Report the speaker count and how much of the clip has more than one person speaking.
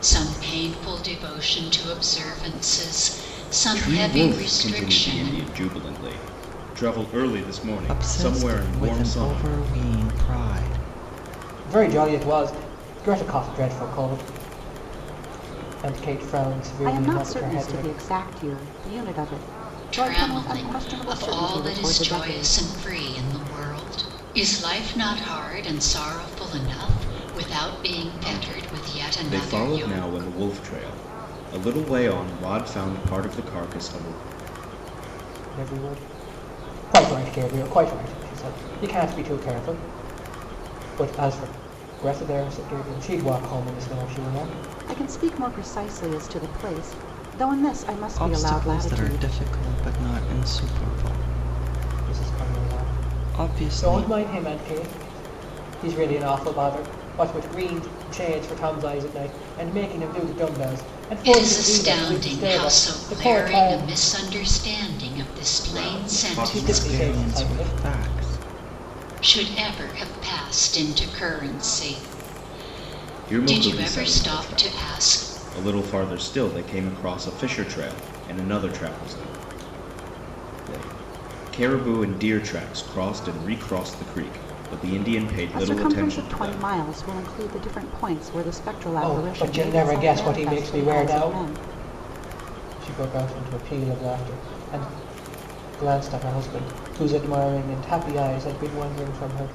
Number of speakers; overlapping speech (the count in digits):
5, about 24%